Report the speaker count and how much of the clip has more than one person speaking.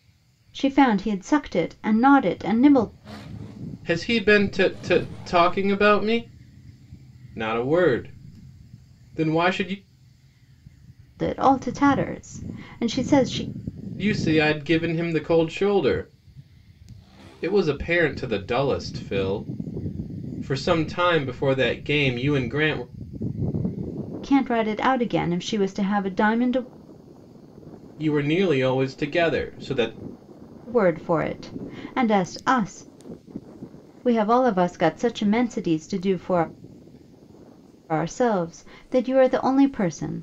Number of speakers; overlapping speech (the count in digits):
2, no overlap